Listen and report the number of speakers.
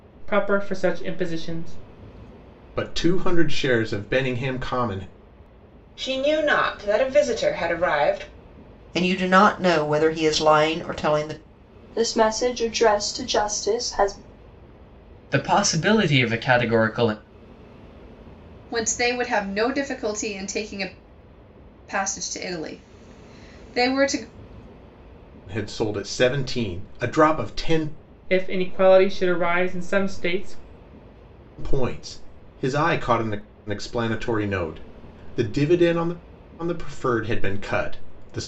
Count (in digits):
7